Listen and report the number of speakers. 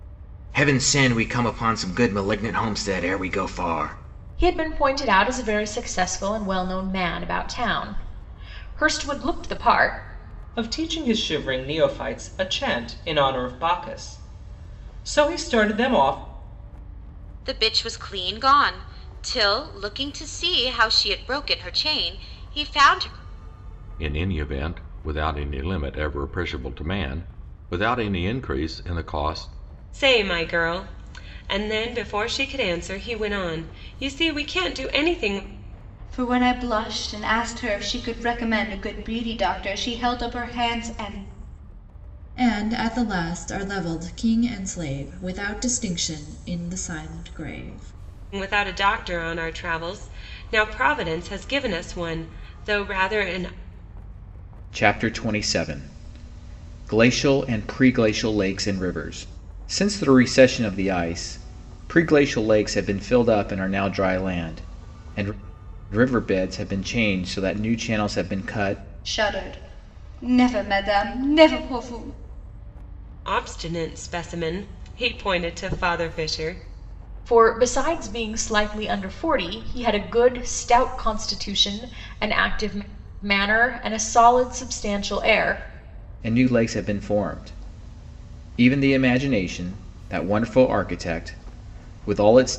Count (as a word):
eight